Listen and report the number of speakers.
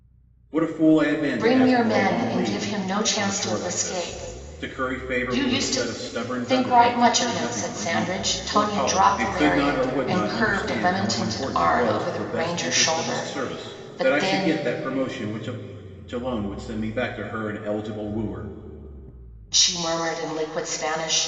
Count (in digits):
2